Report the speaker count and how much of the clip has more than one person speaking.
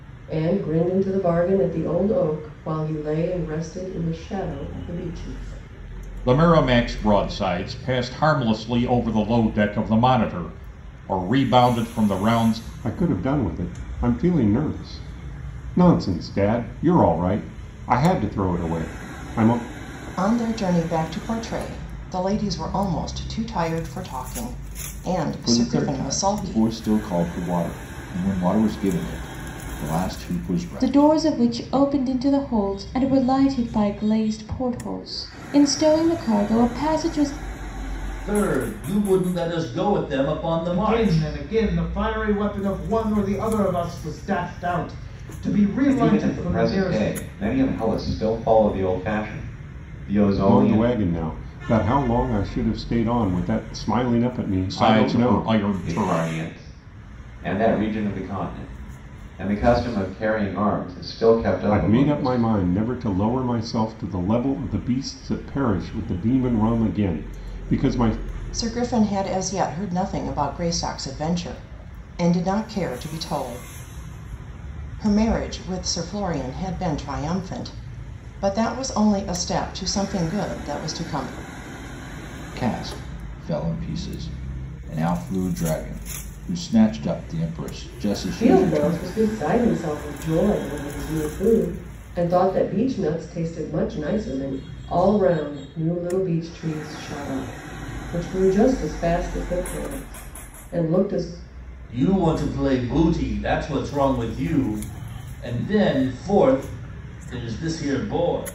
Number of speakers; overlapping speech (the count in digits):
9, about 8%